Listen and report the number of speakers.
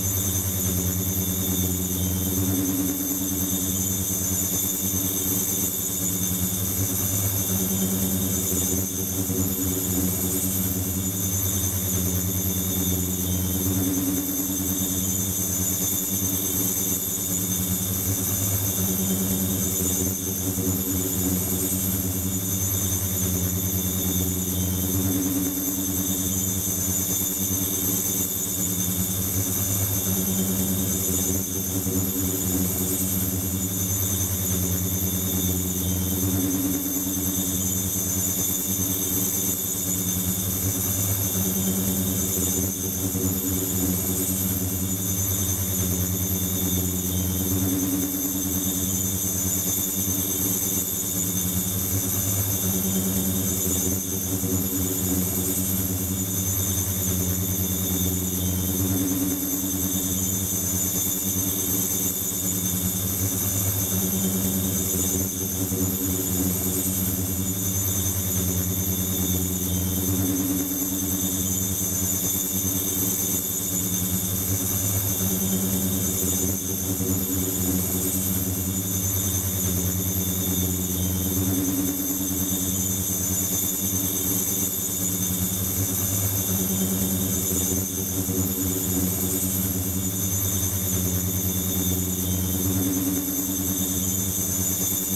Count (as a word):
zero